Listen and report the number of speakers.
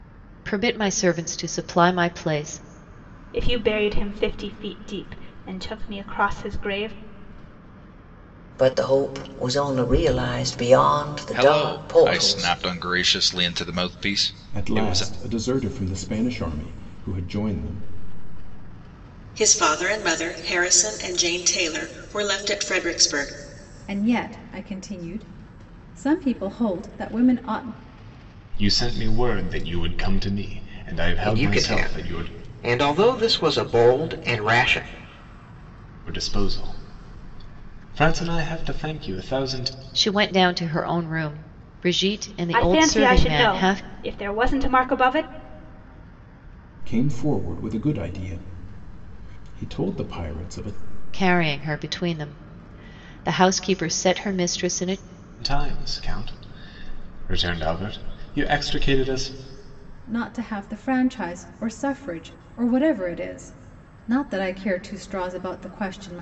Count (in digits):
9